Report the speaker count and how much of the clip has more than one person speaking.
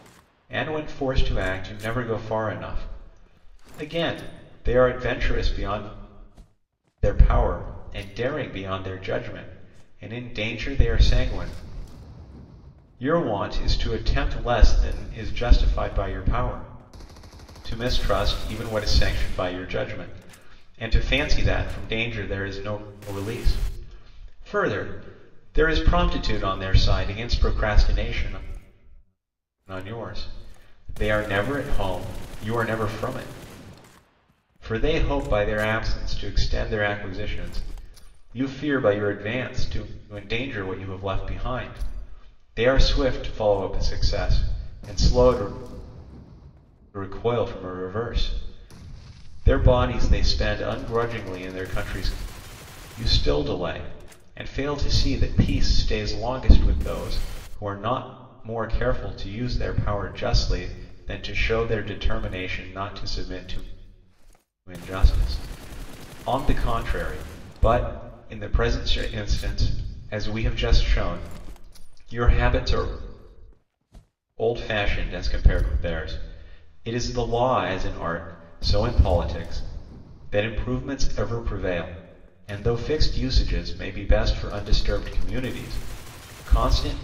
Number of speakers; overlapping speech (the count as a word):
one, no overlap